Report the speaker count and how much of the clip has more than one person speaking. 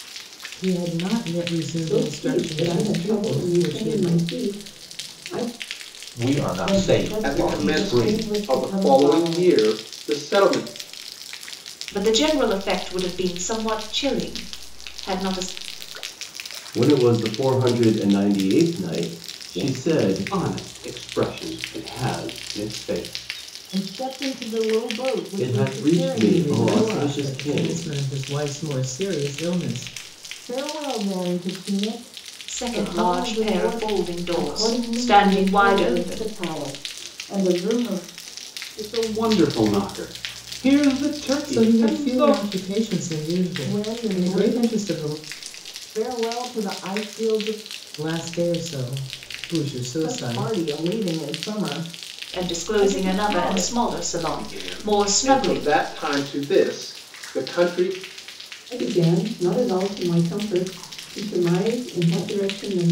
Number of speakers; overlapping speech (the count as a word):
nine, about 29%